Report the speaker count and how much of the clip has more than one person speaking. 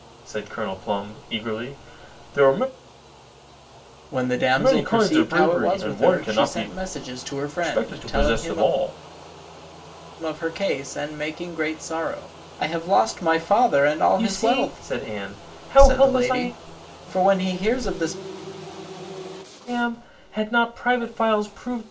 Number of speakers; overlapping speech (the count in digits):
2, about 22%